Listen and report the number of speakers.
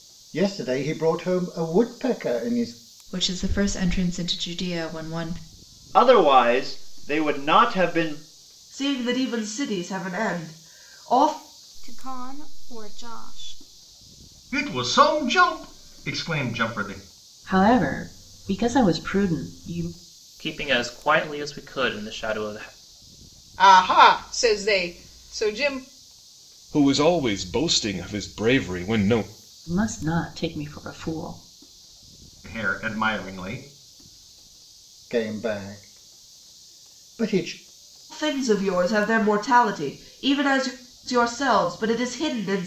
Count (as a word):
ten